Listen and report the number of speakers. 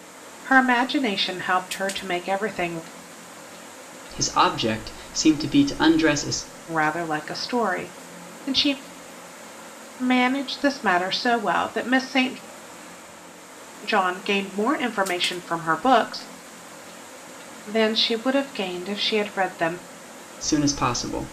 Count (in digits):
2